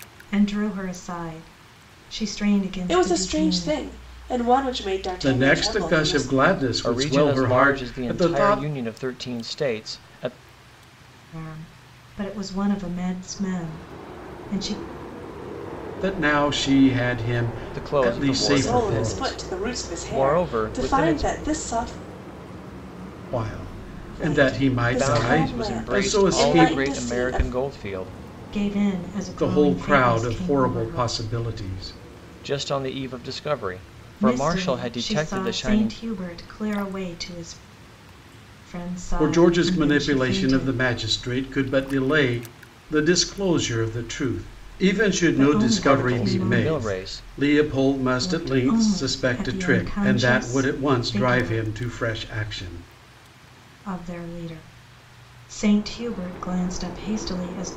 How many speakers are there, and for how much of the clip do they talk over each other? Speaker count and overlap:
four, about 38%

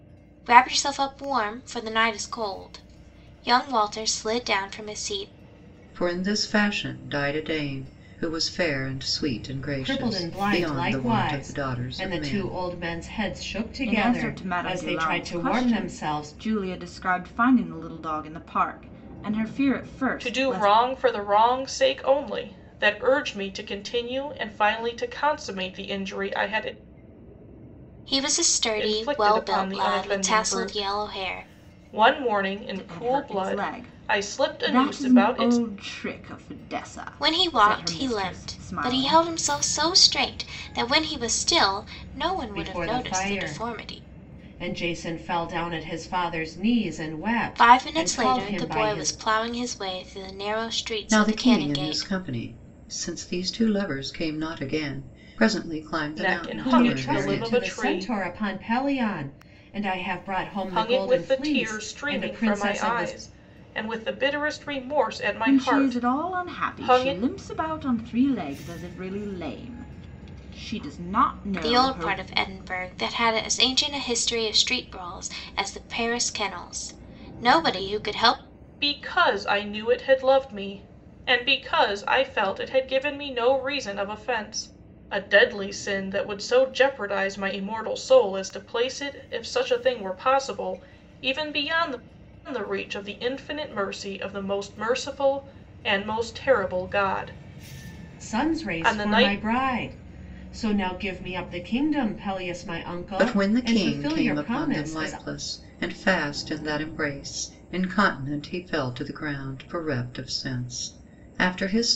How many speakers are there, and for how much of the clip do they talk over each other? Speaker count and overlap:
five, about 26%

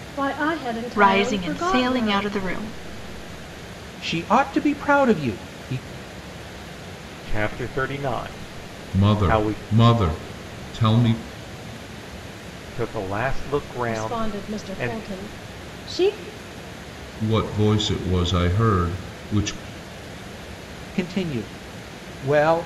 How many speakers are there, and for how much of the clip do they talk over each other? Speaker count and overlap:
five, about 14%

